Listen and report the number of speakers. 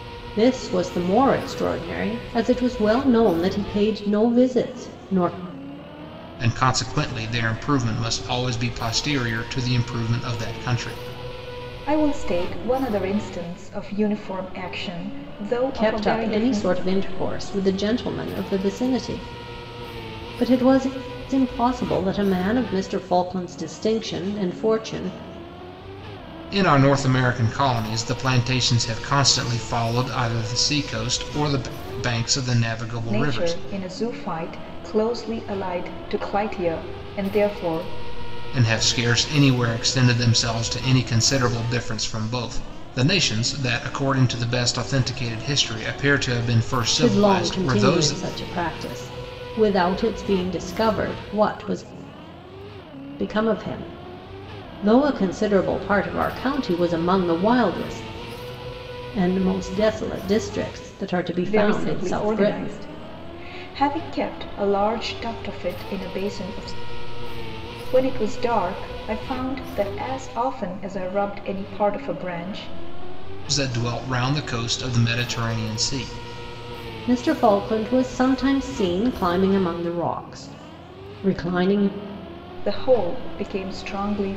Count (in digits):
3